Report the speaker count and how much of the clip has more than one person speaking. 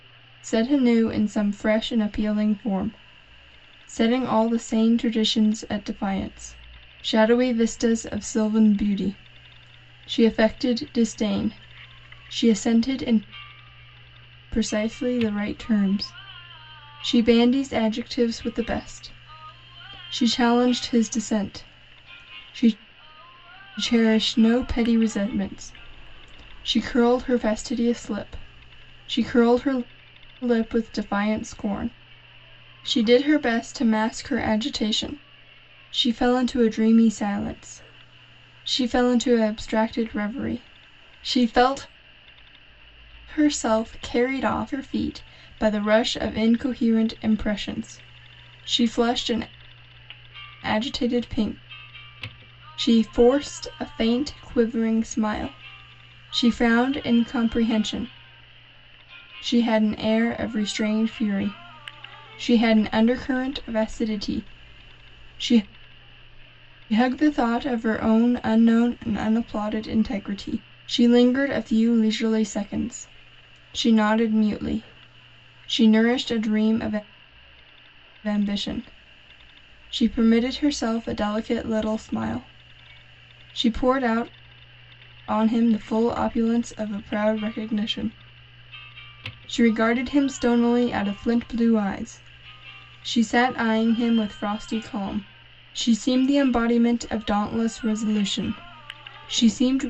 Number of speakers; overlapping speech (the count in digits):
1, no overlap